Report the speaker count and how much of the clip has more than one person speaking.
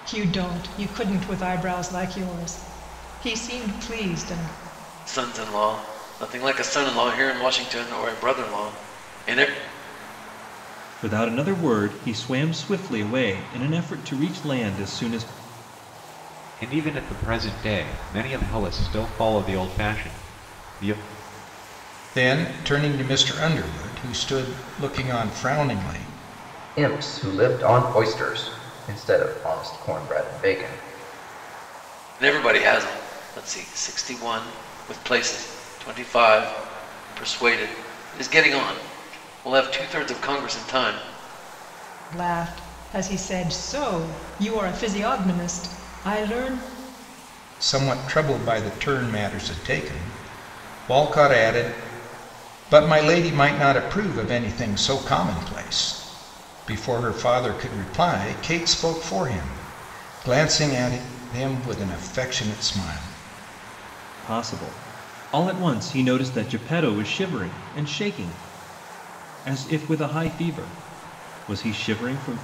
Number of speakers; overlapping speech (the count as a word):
six, no overlap